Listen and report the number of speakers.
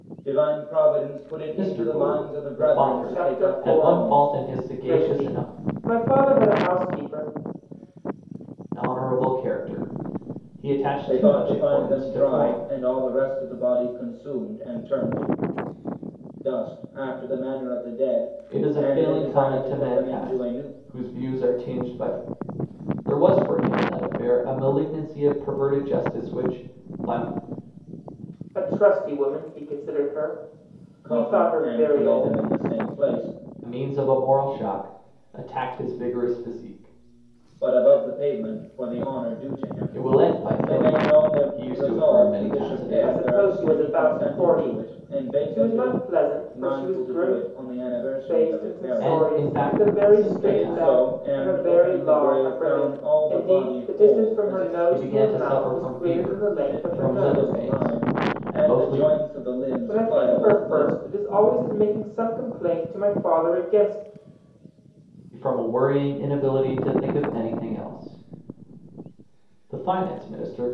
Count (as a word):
three